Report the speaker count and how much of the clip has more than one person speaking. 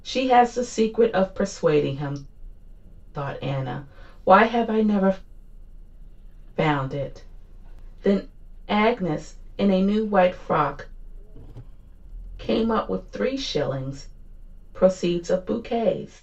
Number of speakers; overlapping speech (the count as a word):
one, no overlap